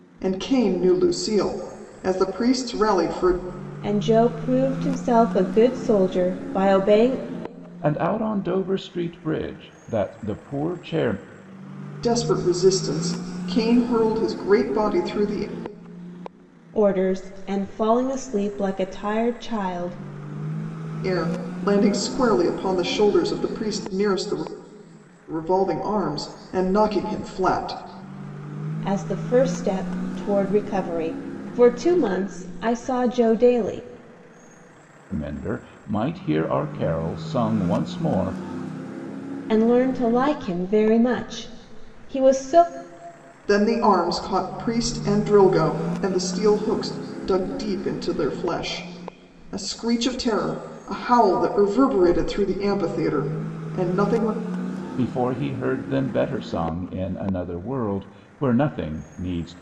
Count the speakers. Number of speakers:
3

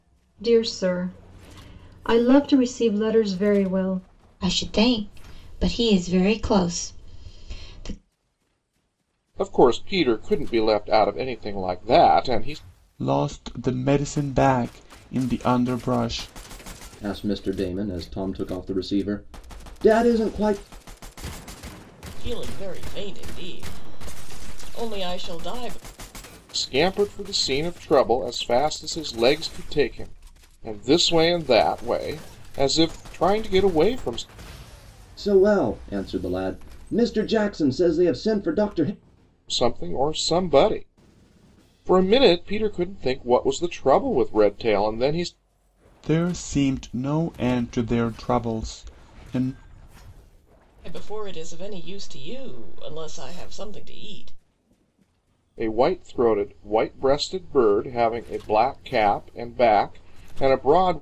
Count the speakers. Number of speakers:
6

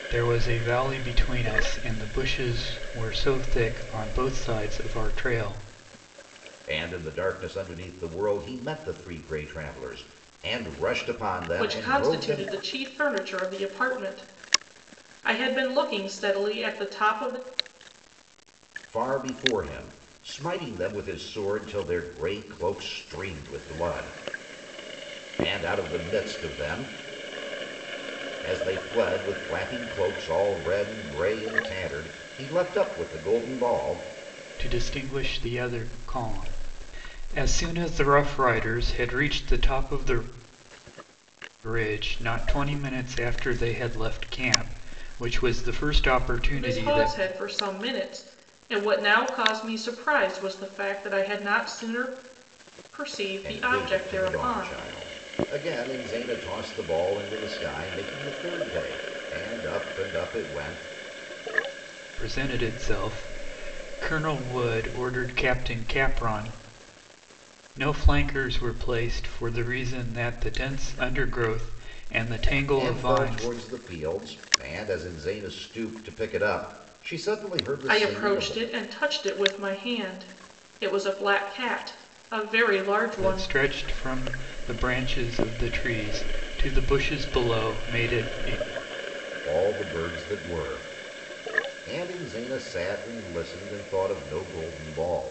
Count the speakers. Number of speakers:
3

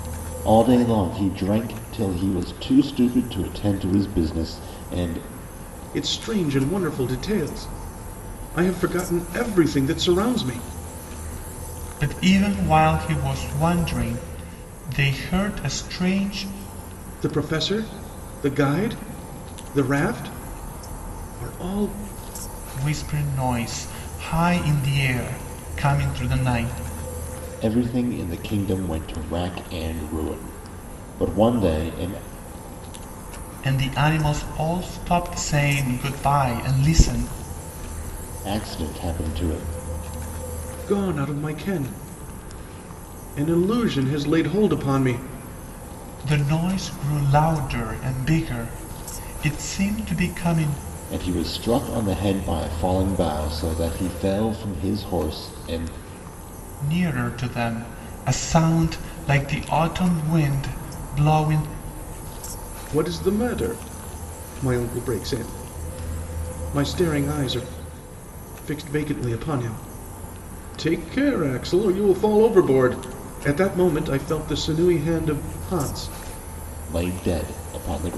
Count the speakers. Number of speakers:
3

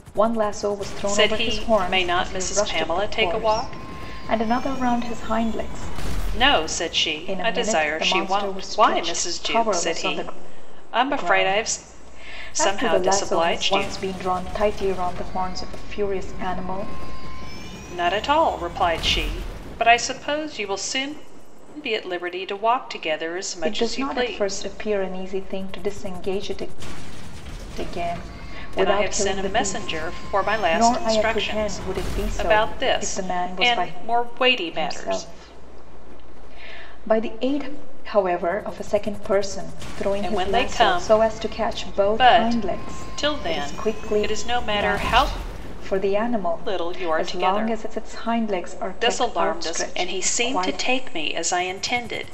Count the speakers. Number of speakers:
2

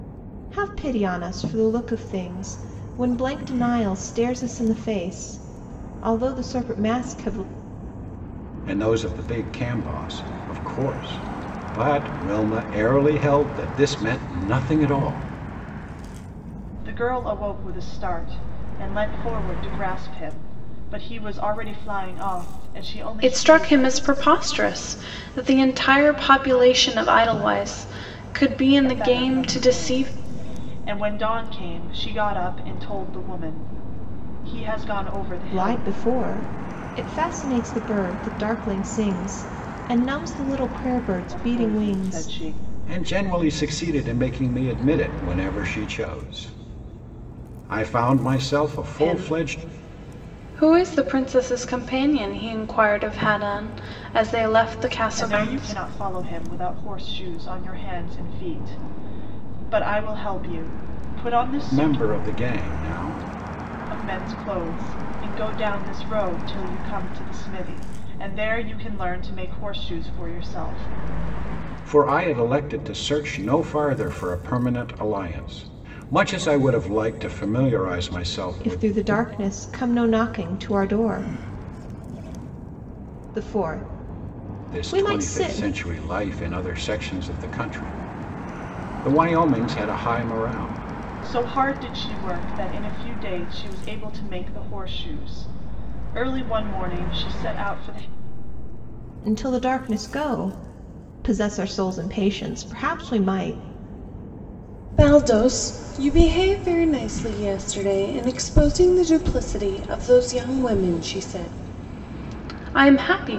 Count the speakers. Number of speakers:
4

